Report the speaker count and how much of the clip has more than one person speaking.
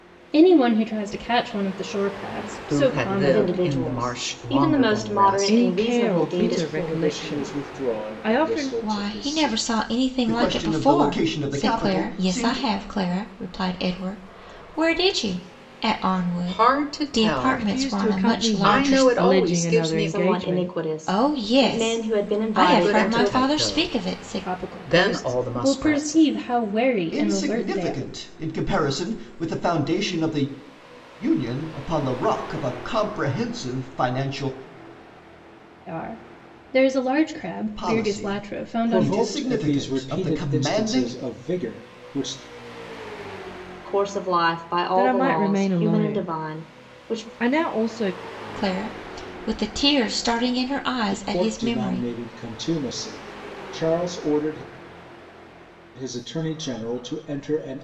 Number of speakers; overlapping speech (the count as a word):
seven, about 46%